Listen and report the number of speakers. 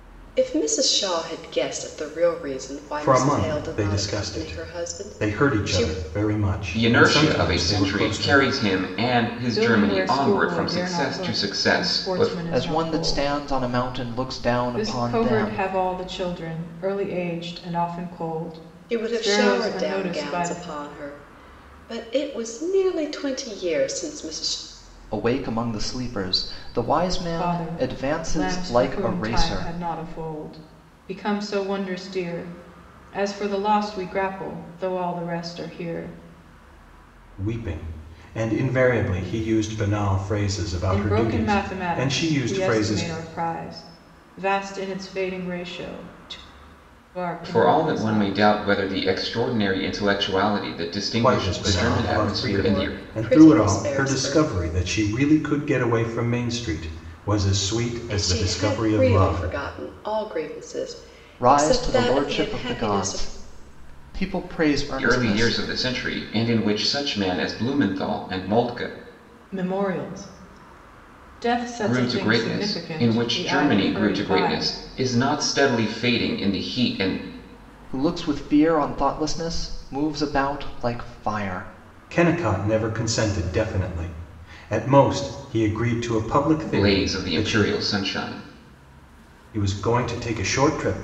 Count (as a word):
five